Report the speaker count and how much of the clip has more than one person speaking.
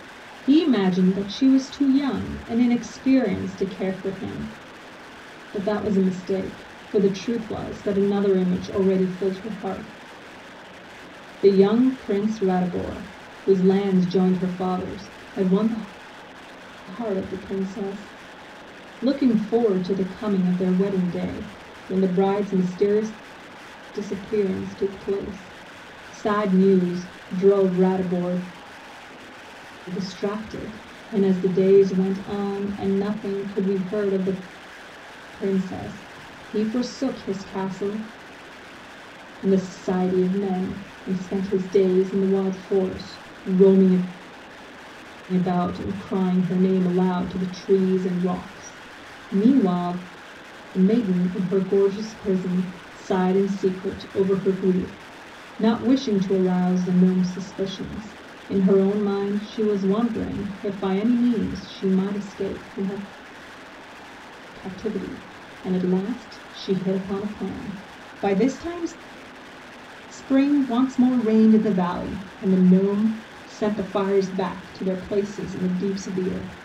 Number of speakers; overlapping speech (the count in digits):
1, no overlap